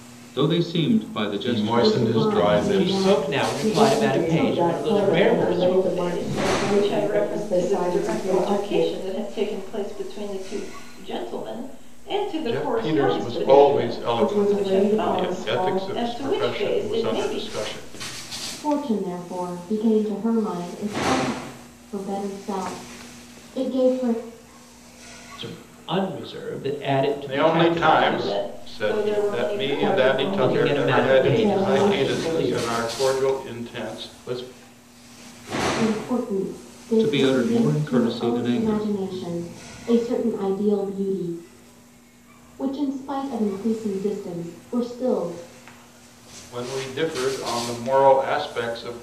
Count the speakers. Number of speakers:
6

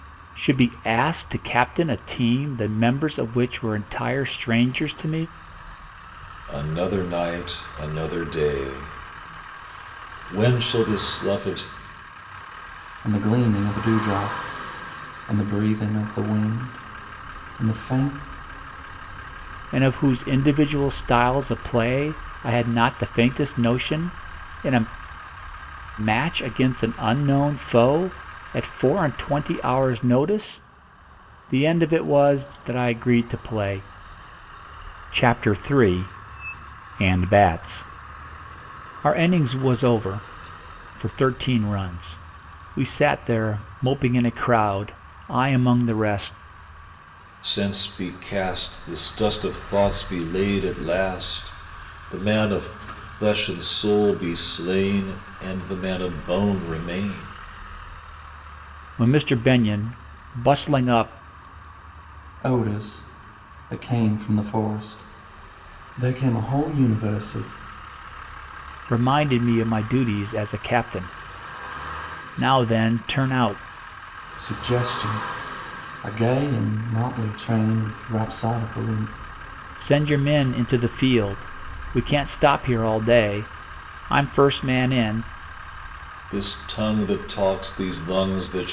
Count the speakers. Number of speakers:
3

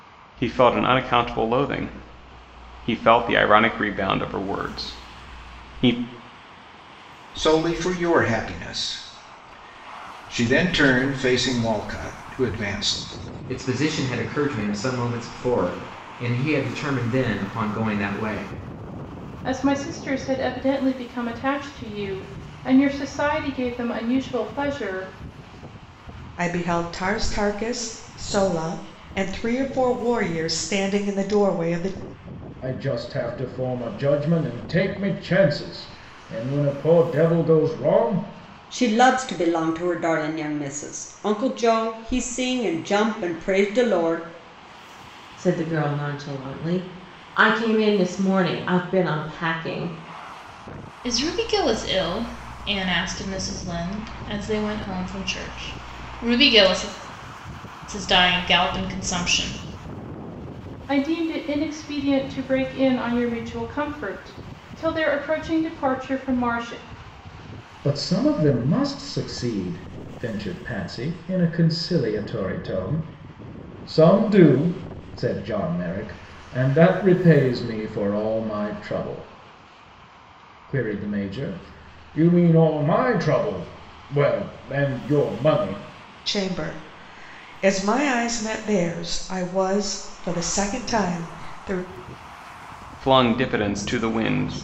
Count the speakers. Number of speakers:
9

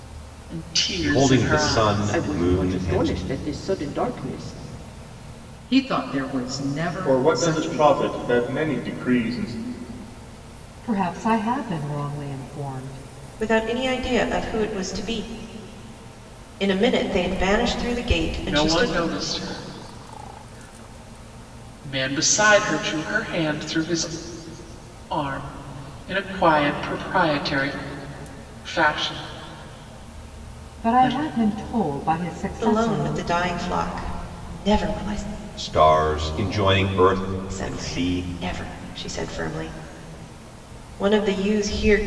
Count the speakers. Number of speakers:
7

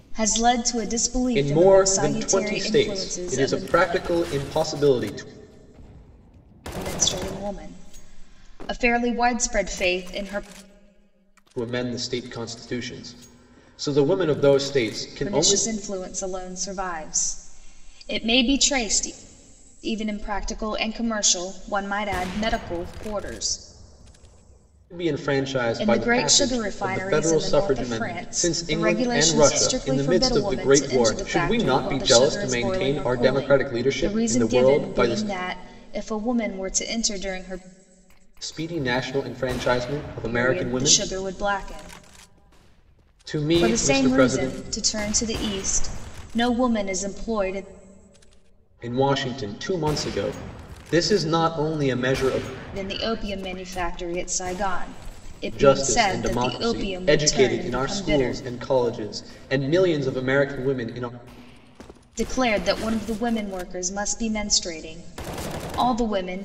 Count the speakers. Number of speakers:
2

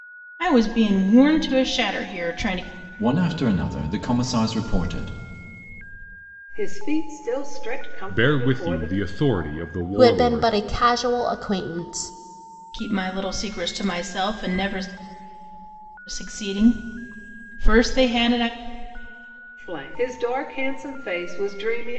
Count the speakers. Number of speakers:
5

